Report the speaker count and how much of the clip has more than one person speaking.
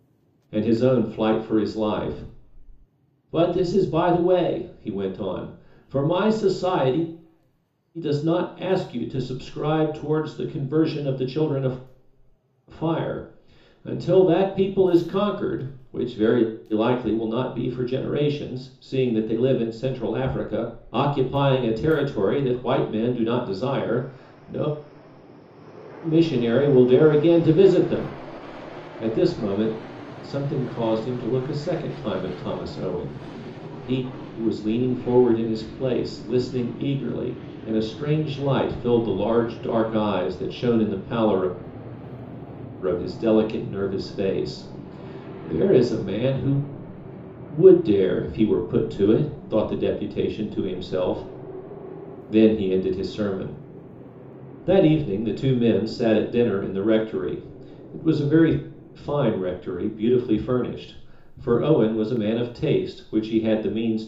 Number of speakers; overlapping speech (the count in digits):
1, no overlap